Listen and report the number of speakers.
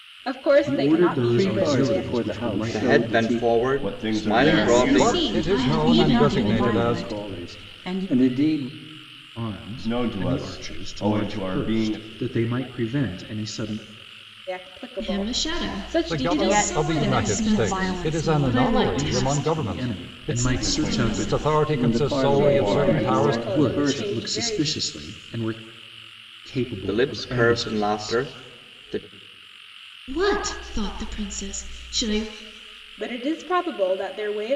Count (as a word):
eight